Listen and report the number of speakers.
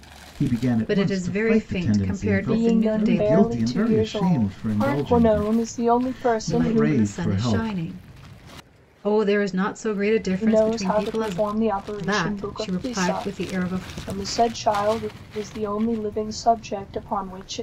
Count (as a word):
three